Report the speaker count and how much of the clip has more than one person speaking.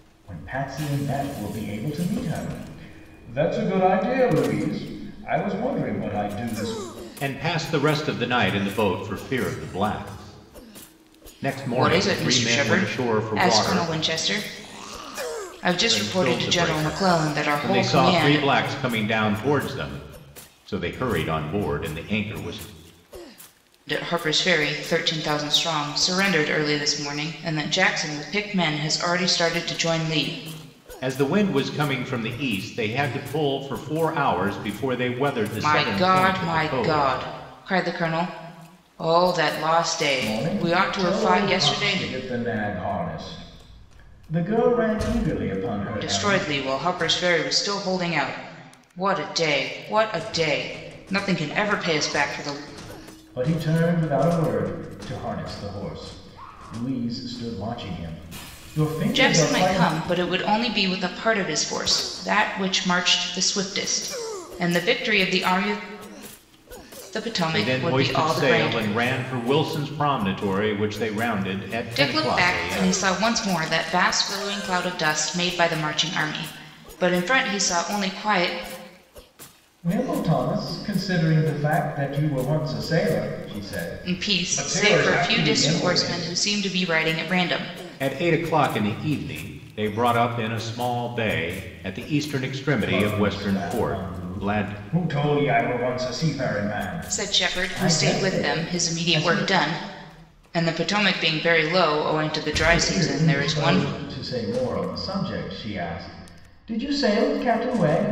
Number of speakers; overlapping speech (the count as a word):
three, about 19%